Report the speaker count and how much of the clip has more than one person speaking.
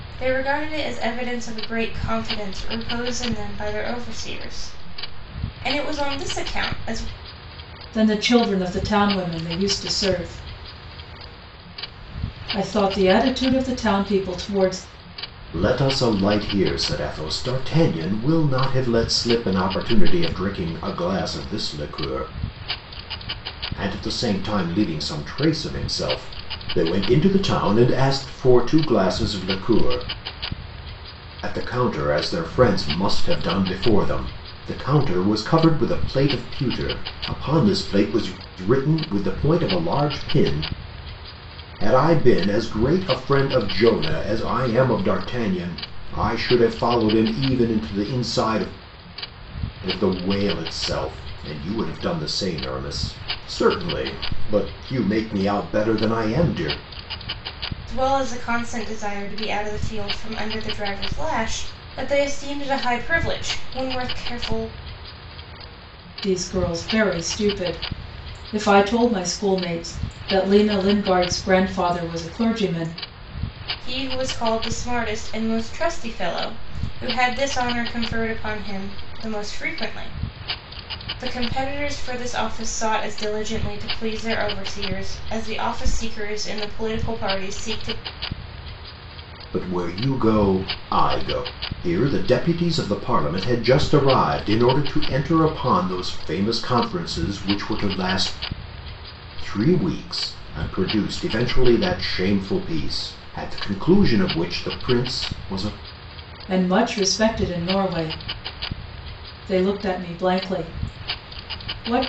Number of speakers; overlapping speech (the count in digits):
3, no overlap